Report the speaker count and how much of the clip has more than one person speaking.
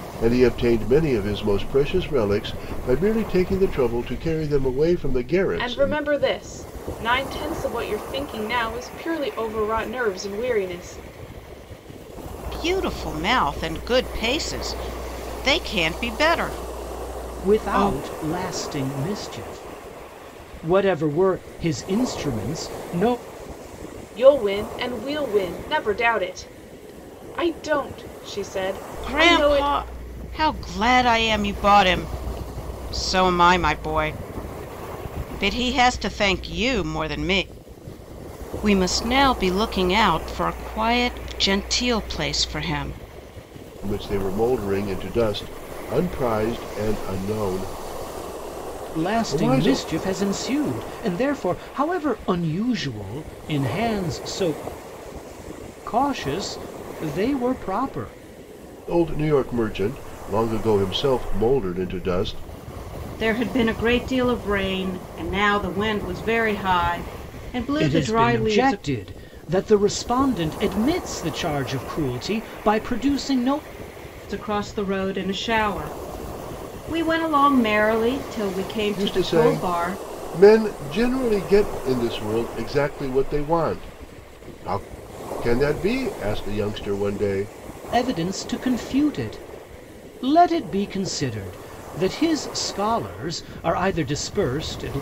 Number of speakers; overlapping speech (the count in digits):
4, about 5%